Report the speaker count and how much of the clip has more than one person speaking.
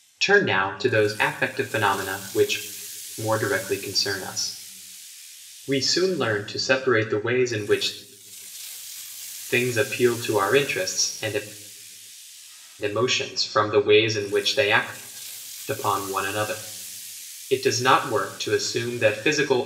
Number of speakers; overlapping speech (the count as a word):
one, no overlap